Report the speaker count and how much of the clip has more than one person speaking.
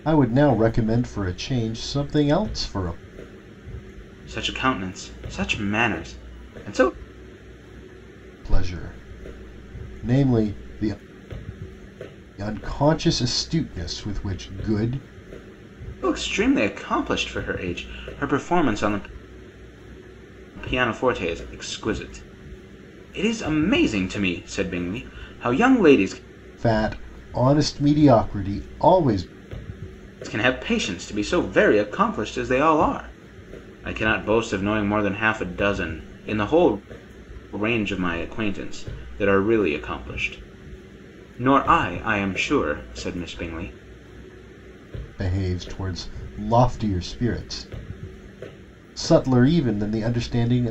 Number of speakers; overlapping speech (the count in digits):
2, no overlap